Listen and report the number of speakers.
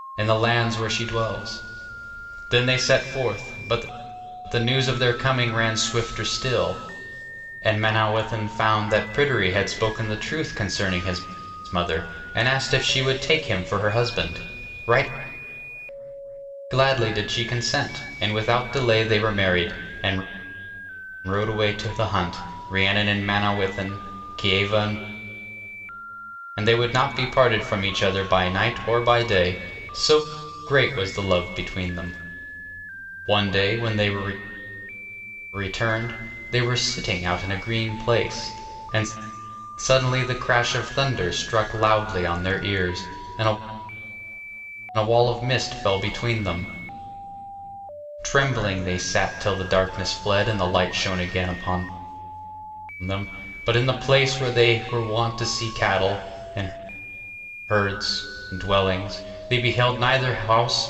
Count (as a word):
one